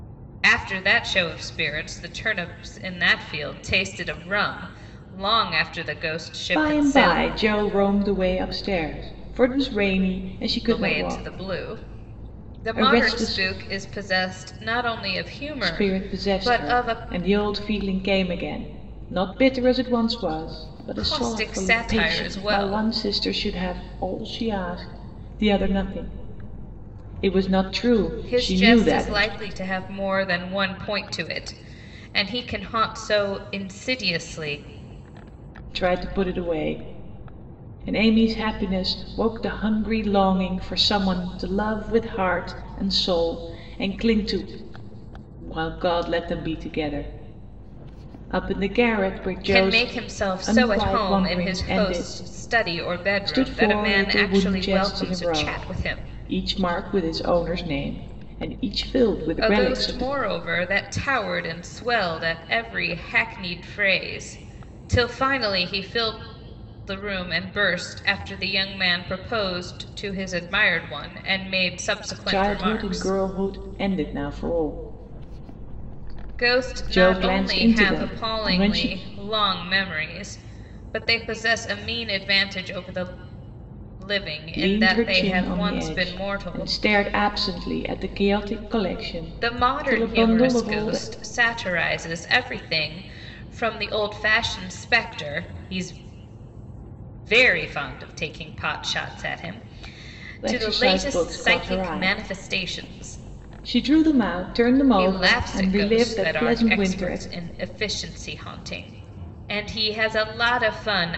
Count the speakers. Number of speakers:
two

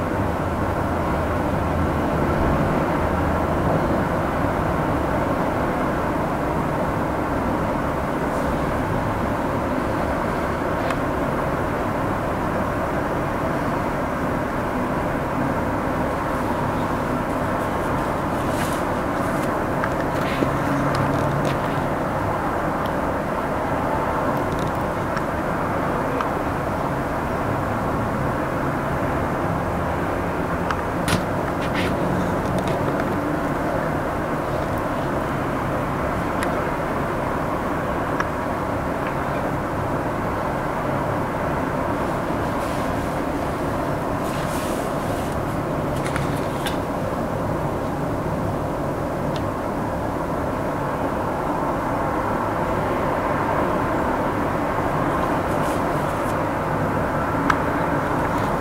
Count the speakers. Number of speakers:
zero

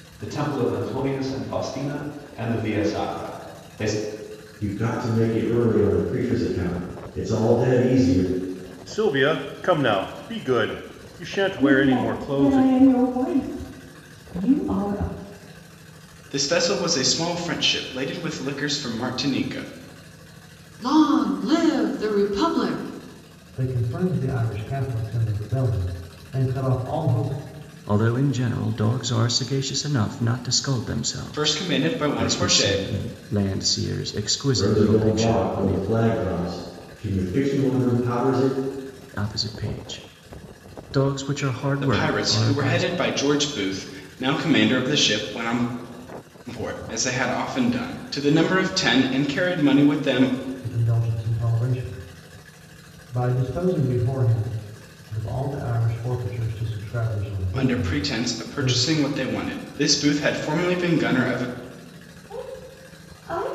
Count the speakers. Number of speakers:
eight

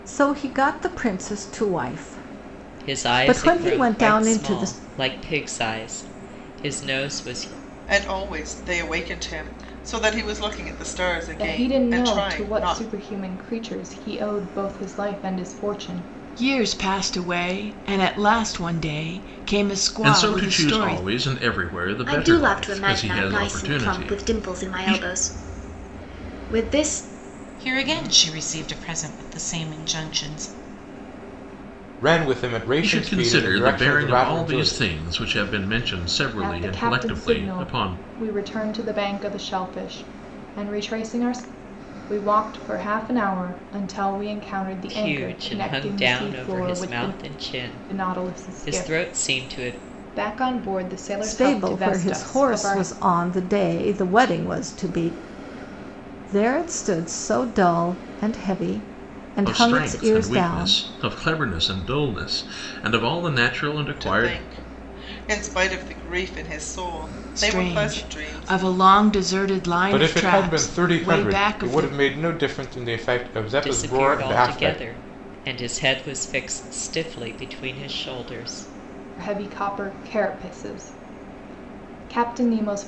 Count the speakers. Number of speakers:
nine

